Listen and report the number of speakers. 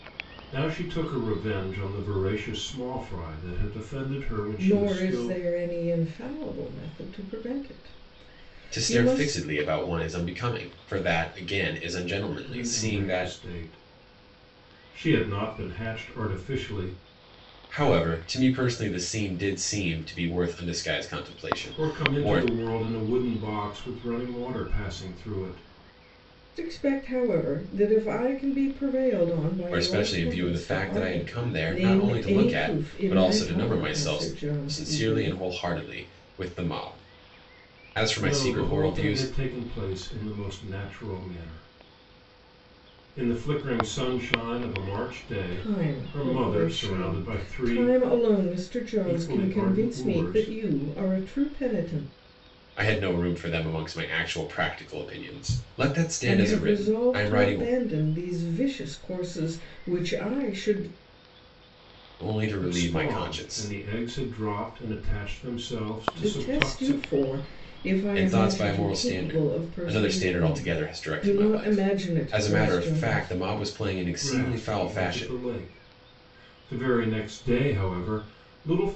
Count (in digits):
3